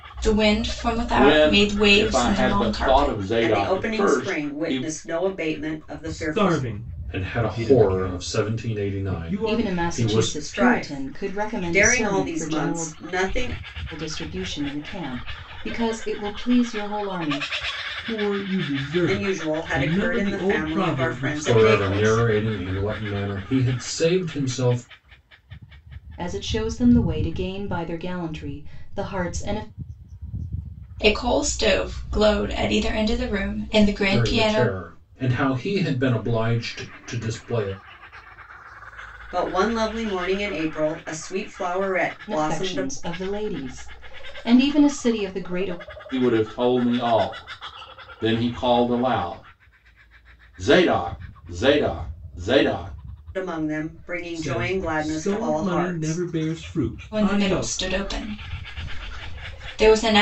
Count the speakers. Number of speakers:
six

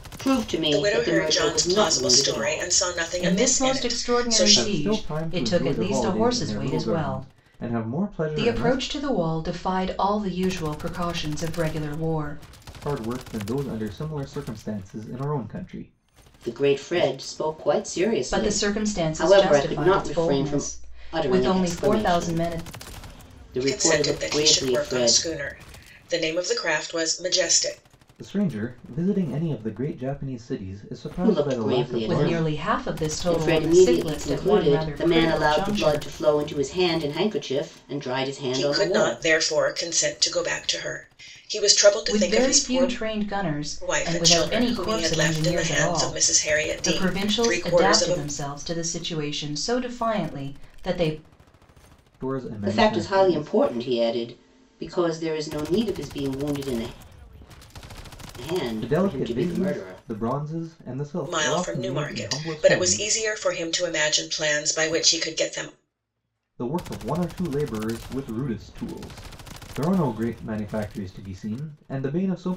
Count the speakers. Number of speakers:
four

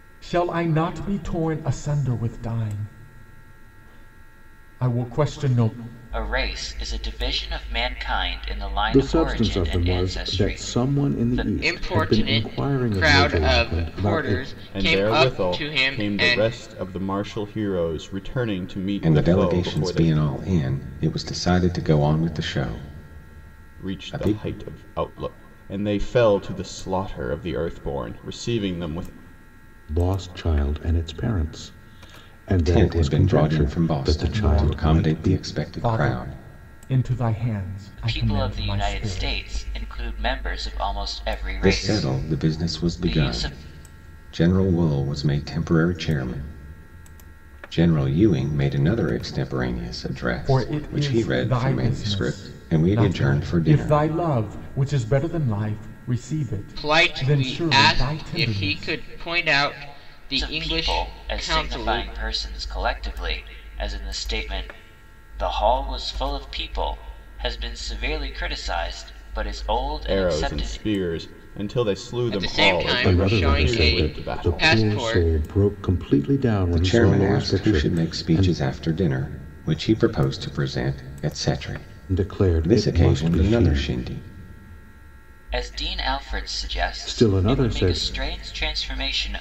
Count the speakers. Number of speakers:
six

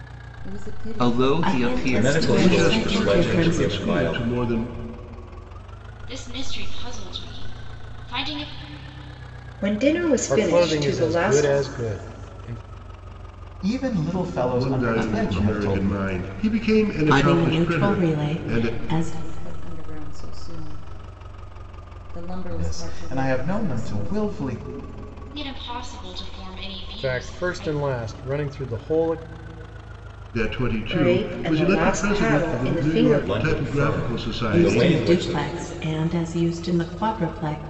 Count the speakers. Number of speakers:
nine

